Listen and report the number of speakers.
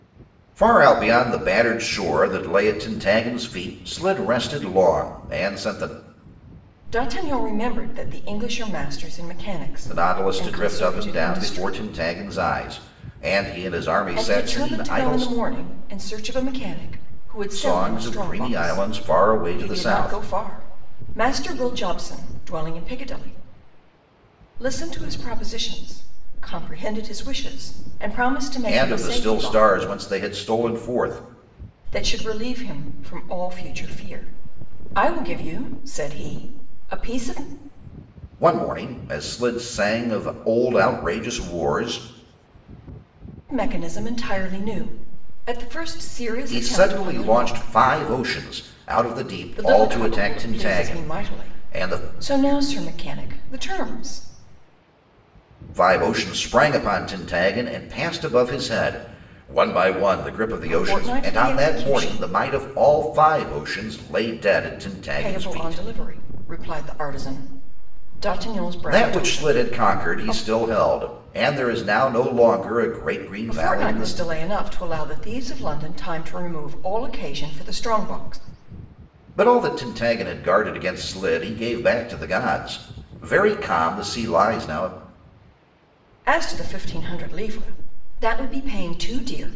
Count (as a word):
two